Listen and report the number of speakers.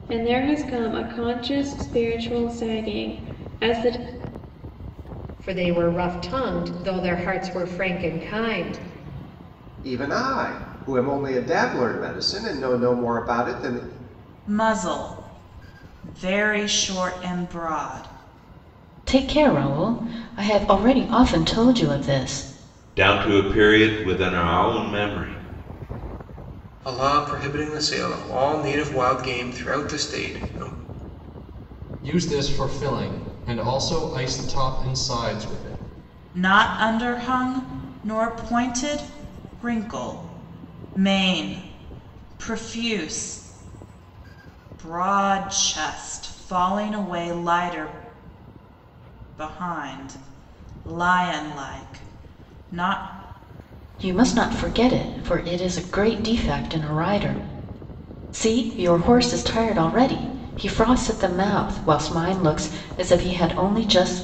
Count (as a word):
eight